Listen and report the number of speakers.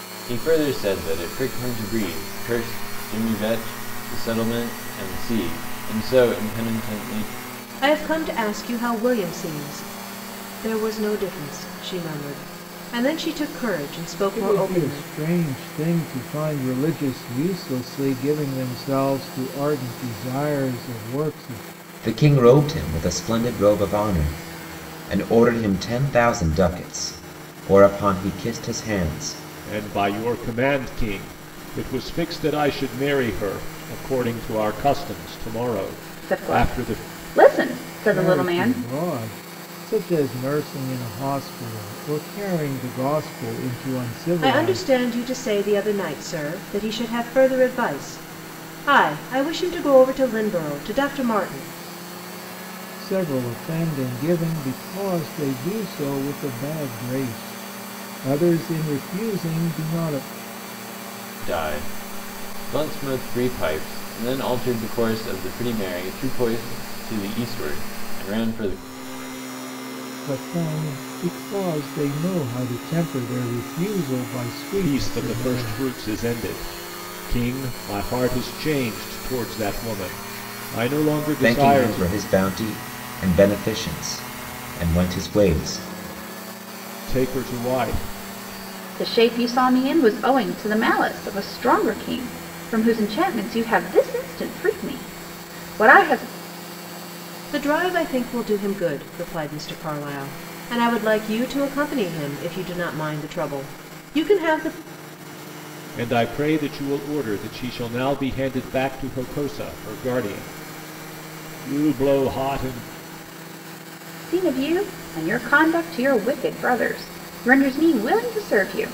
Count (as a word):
six